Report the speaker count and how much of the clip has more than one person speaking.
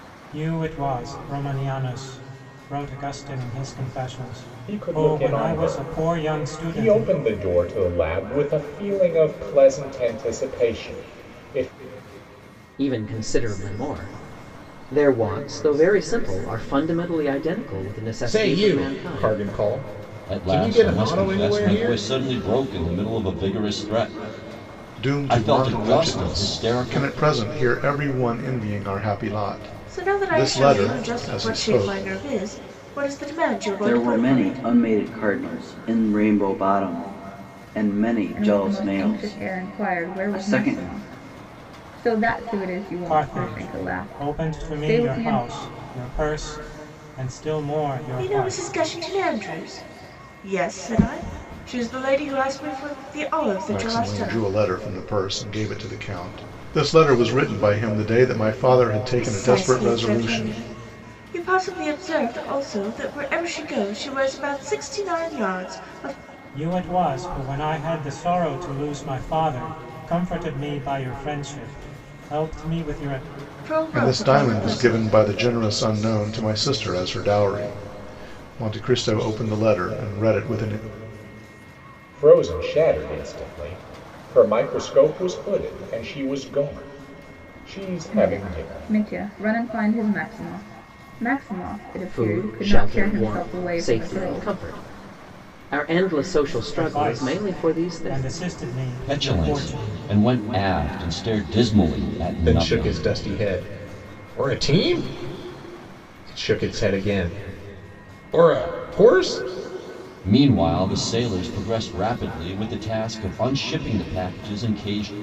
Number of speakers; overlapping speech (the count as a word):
nine, about 23%